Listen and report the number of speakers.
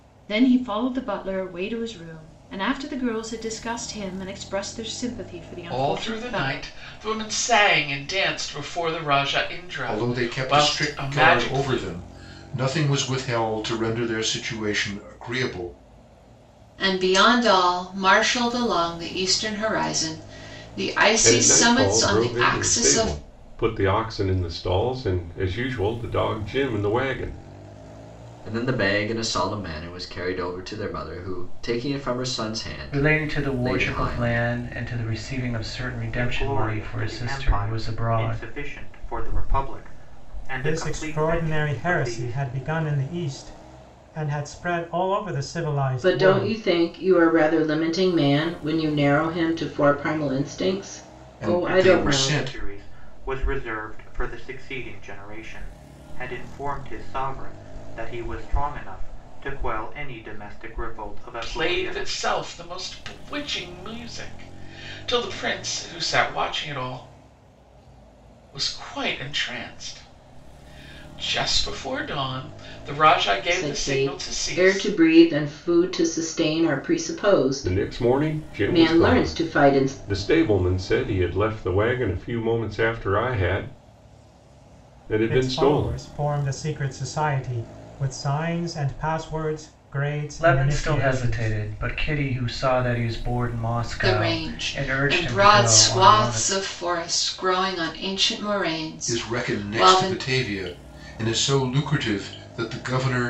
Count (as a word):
ten